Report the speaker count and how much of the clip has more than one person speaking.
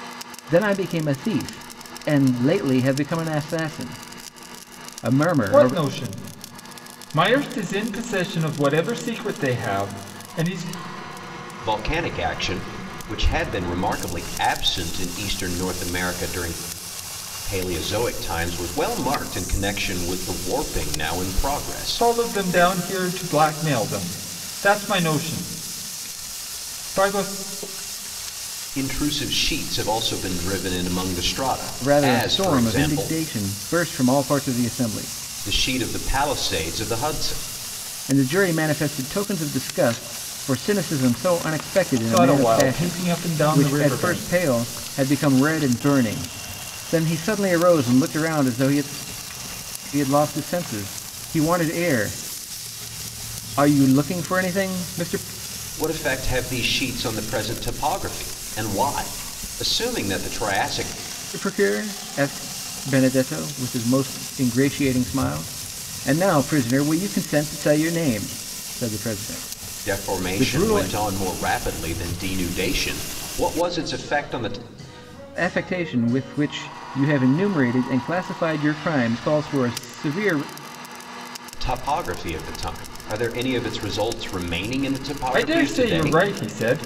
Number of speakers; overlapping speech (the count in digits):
3, about 7%